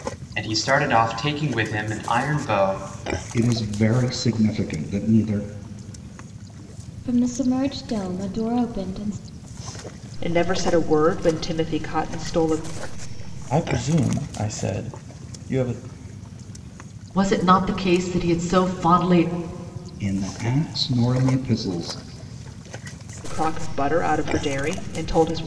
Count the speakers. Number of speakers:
six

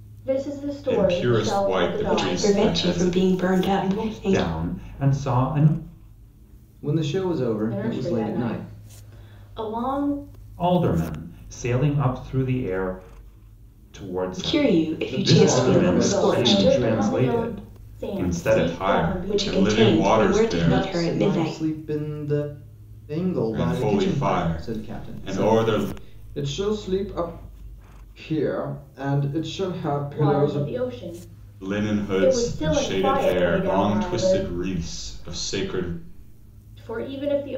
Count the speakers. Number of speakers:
five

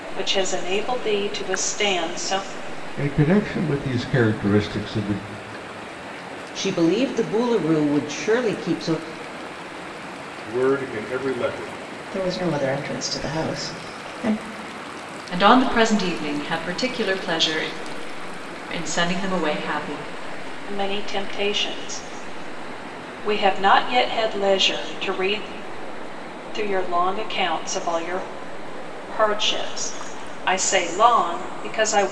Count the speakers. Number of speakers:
six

